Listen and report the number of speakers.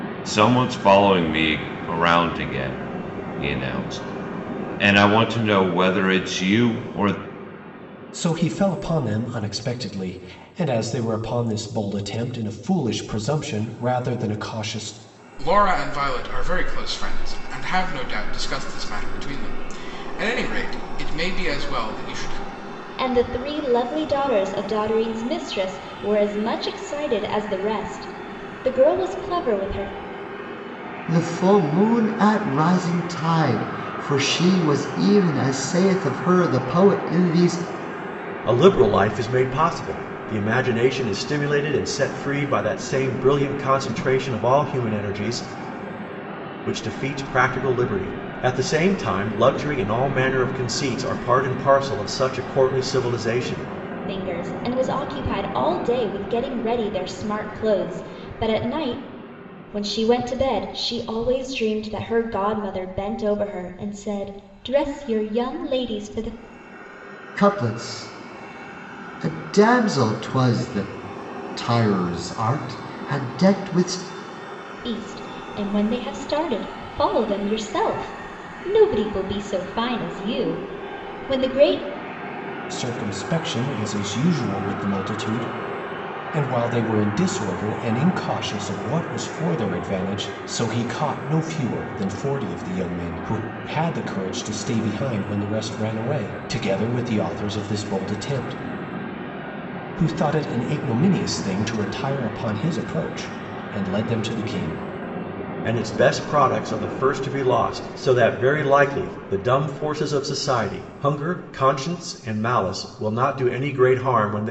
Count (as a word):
six